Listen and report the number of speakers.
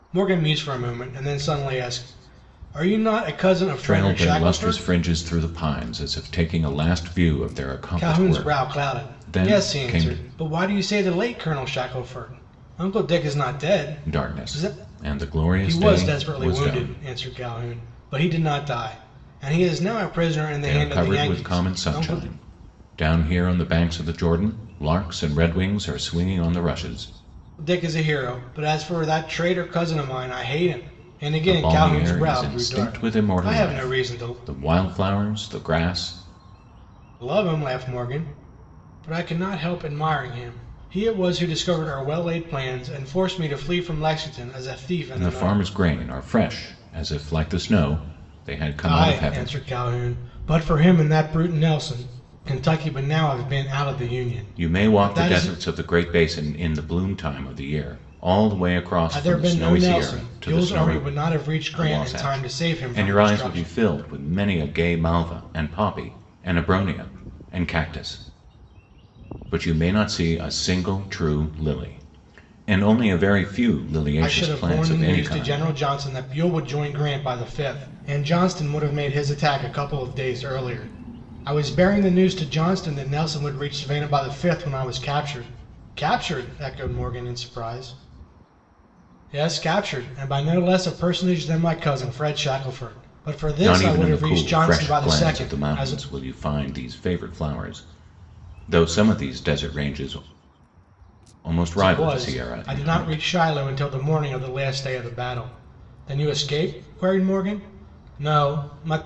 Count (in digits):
2